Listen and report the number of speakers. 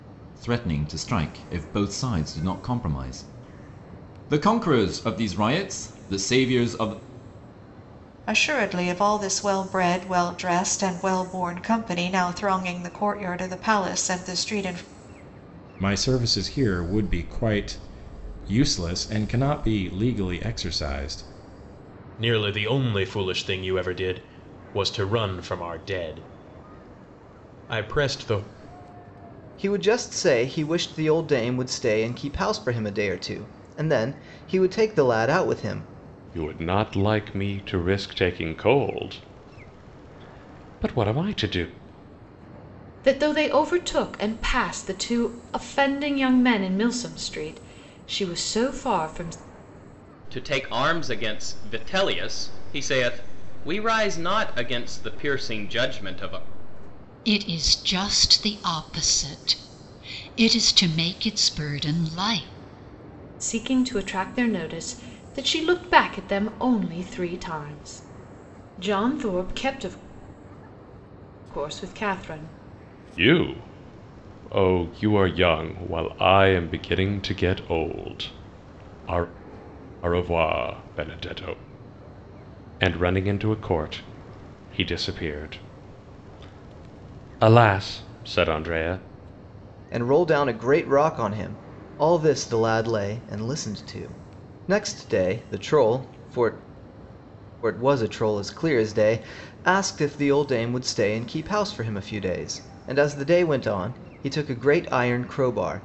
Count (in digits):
9